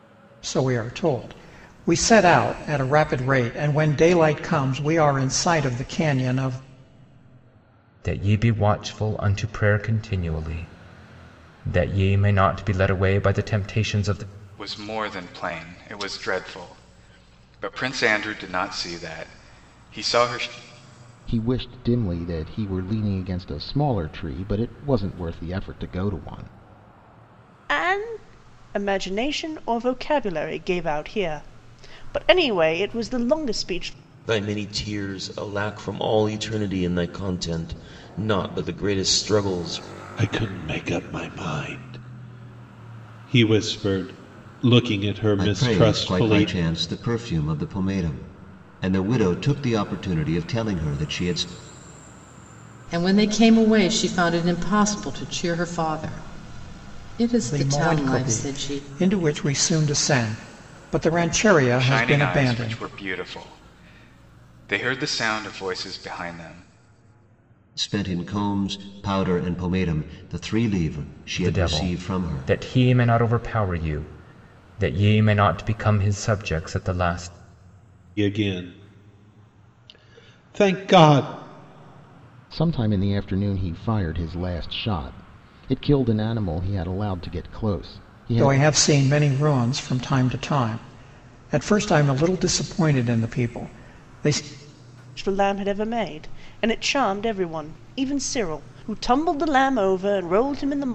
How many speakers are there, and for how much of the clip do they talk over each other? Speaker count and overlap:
nine, about 5%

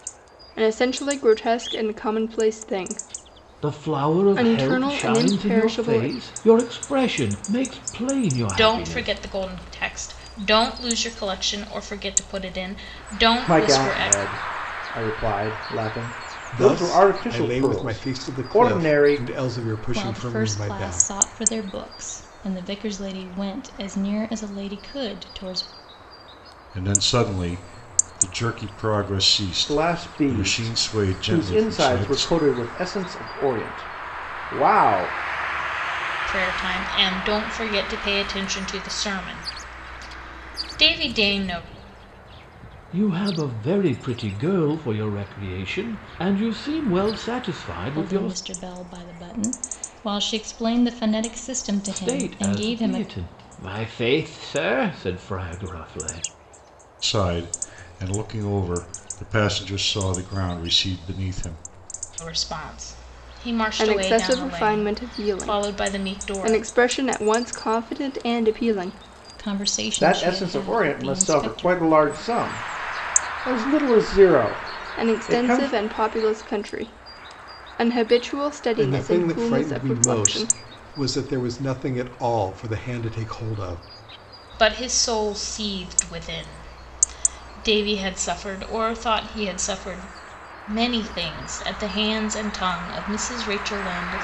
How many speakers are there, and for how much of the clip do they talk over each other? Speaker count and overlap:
seven, about 22%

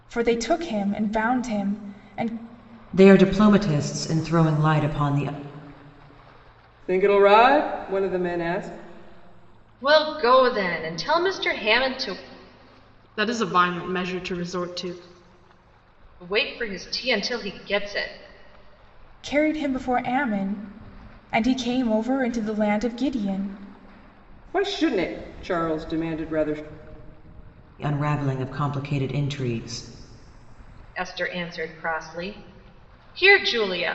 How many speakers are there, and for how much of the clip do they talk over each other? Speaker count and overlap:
five, no overlap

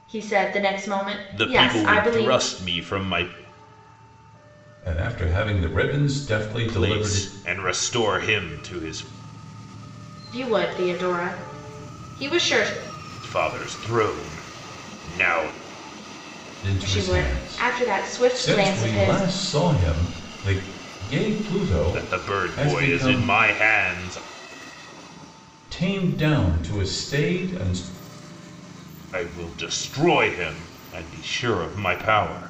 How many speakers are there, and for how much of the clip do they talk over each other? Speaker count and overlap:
three, about 15%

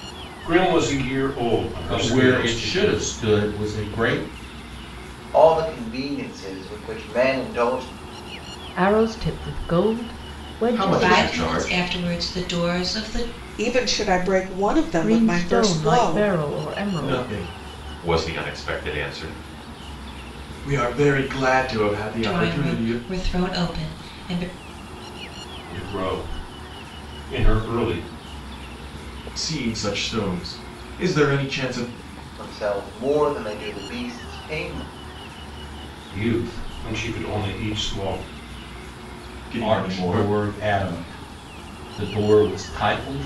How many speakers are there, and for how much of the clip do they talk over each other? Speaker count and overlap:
seven, about 13%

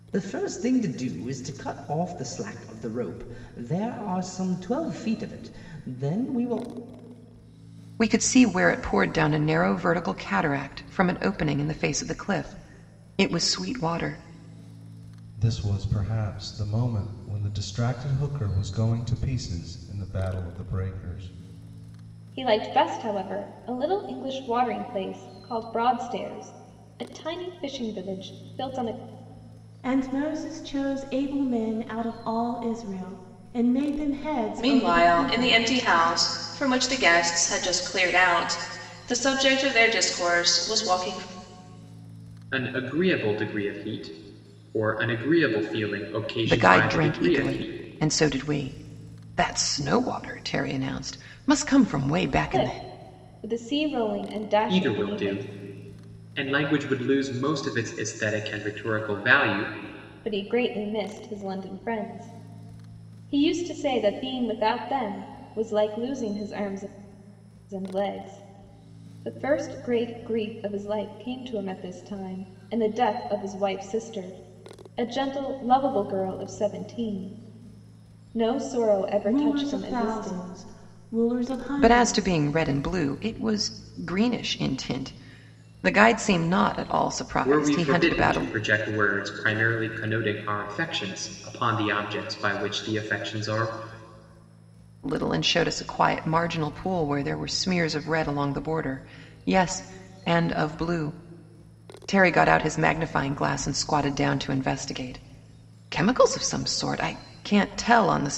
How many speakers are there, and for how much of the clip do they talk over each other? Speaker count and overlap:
seven, about 6%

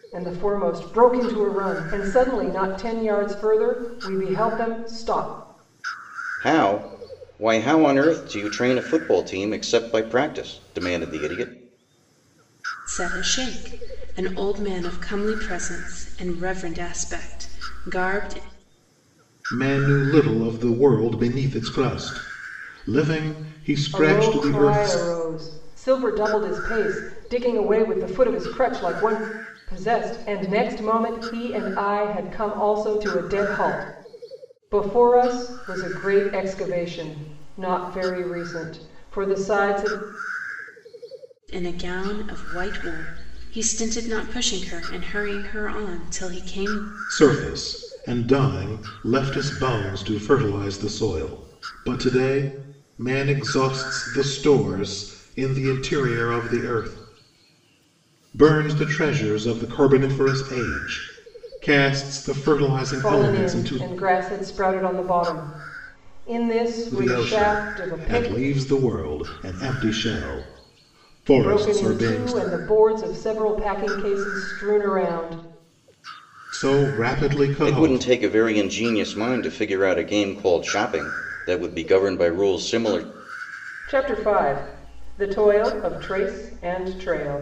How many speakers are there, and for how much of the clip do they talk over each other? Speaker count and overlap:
four, about 6%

